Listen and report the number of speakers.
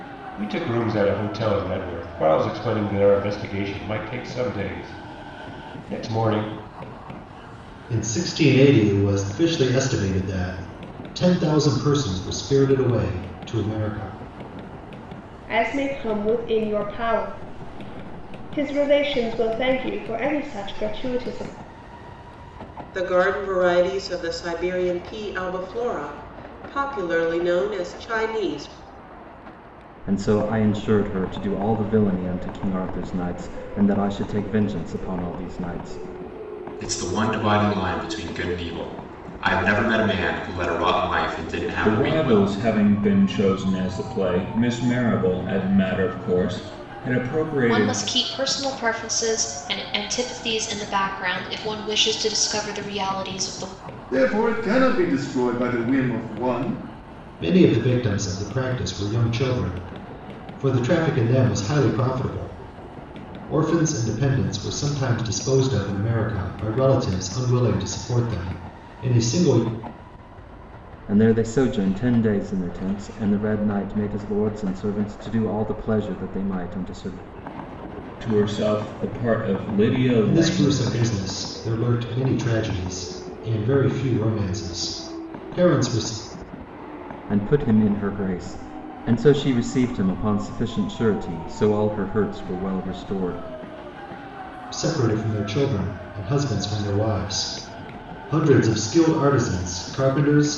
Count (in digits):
9